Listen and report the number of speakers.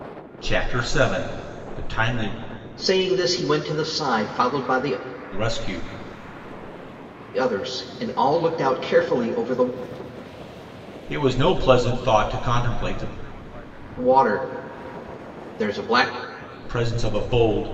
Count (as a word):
two